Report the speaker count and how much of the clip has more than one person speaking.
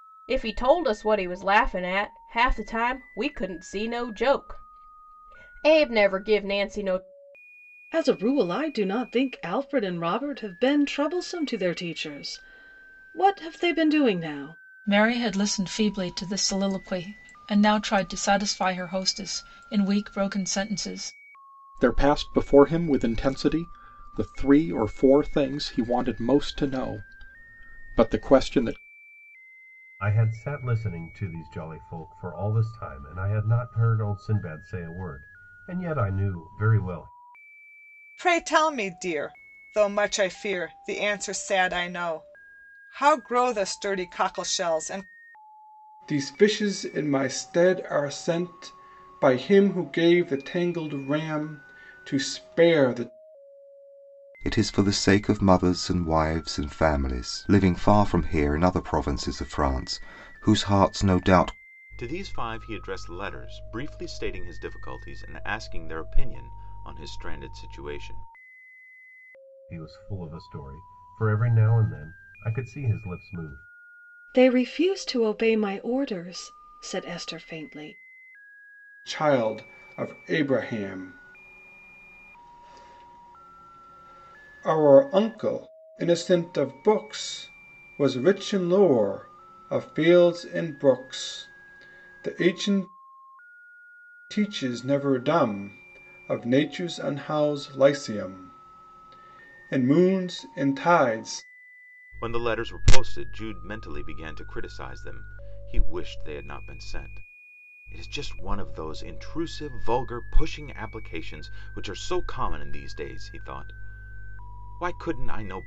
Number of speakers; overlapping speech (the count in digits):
9, no overlap